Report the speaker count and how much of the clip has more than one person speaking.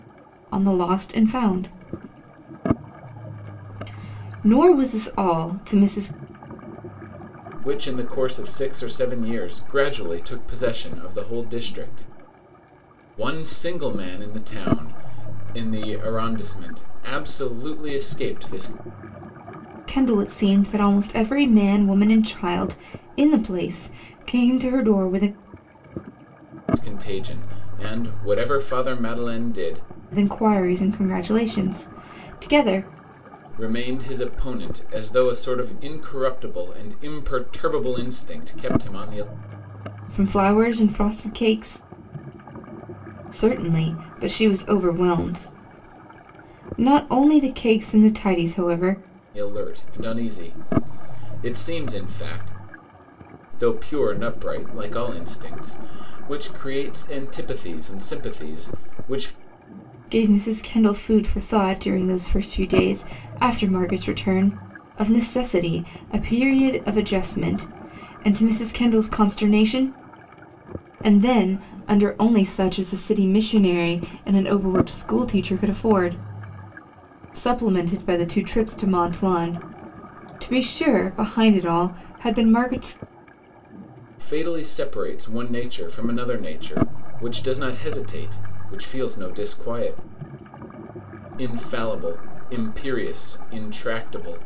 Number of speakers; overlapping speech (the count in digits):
2, no overlap